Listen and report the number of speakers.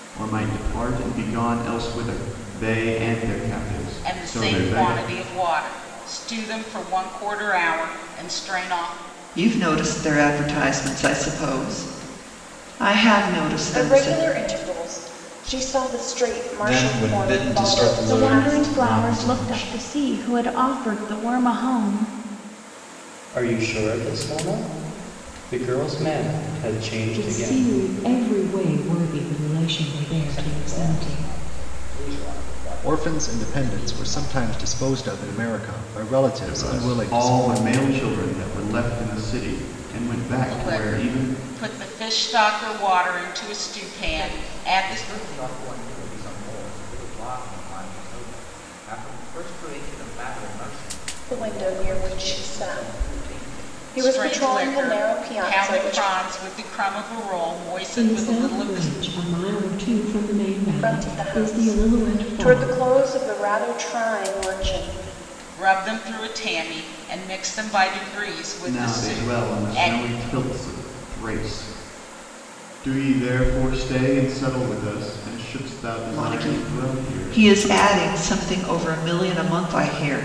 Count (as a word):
ten